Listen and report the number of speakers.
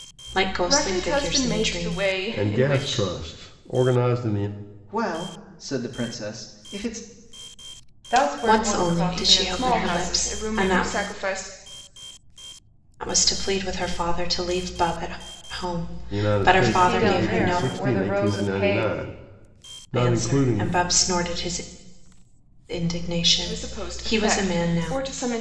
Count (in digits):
5